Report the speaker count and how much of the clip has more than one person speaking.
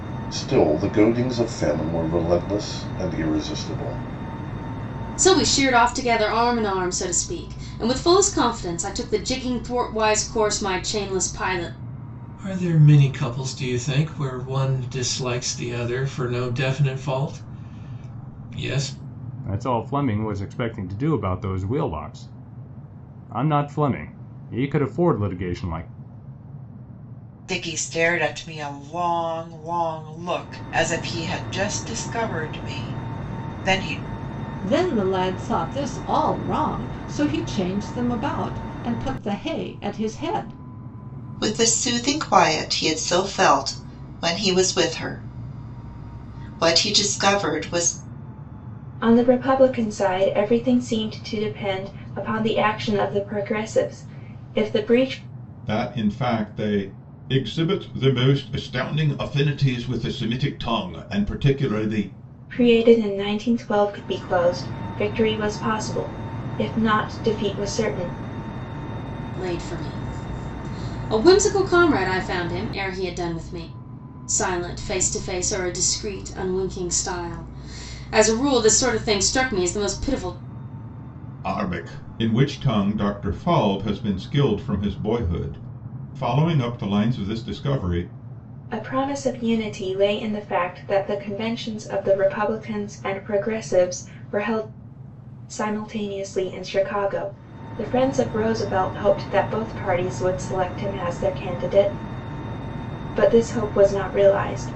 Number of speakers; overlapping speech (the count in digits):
9, no overlap